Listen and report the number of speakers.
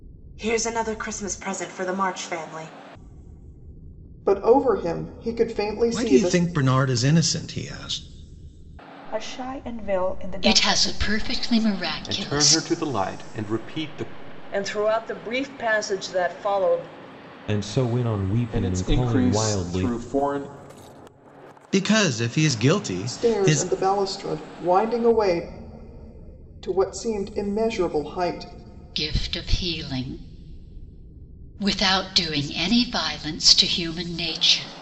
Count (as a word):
nine